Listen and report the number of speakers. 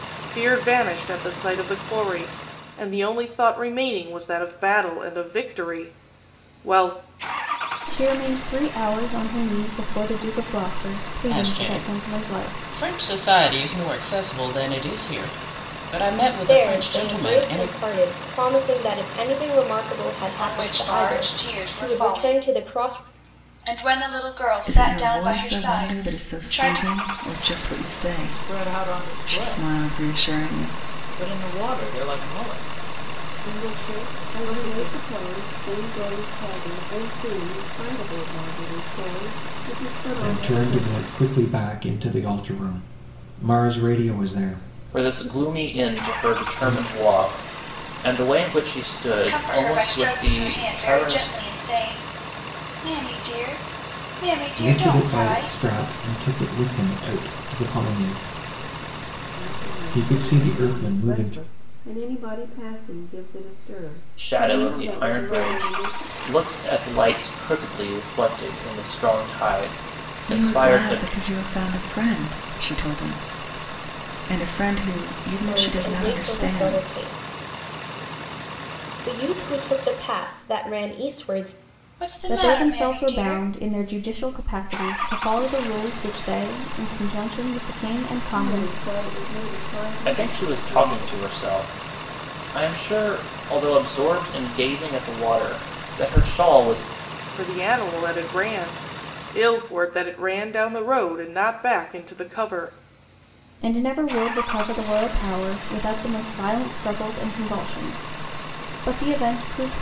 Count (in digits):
10